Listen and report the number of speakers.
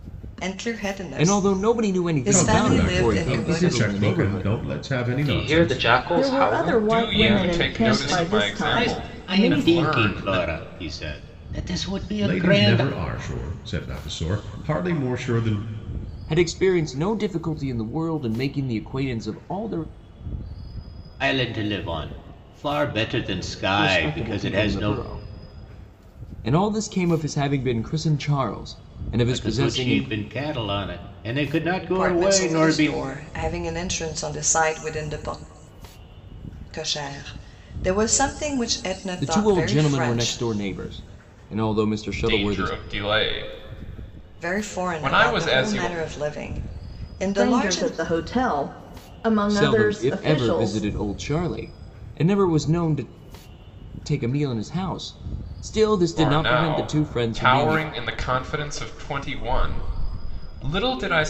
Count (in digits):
7